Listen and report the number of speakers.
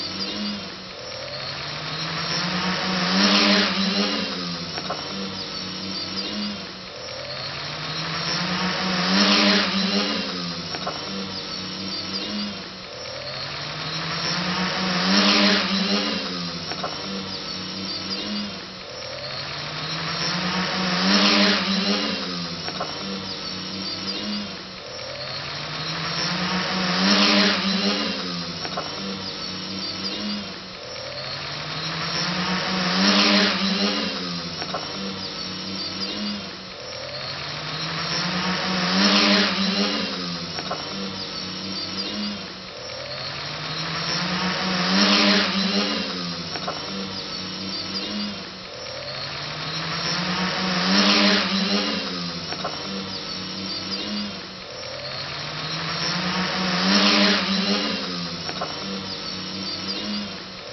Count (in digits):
0